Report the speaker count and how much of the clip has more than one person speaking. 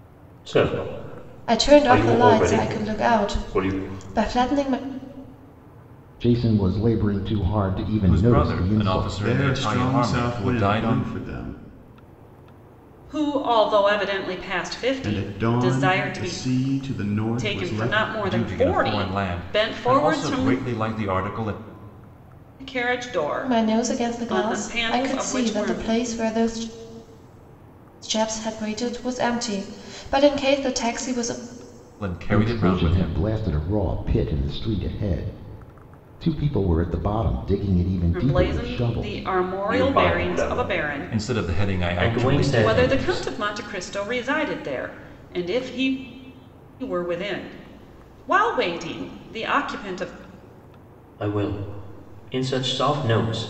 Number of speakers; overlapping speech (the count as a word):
six, about 34%